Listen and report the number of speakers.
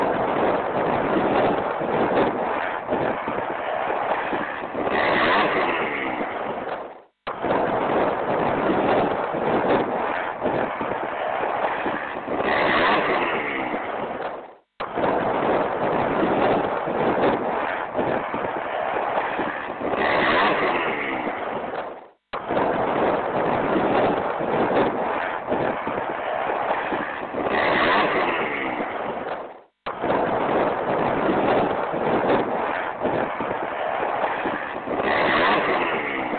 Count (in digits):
0